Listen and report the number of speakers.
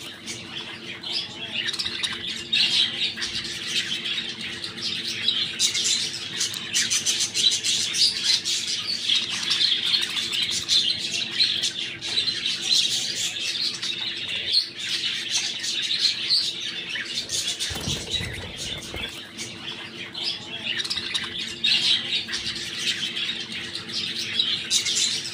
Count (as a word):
zero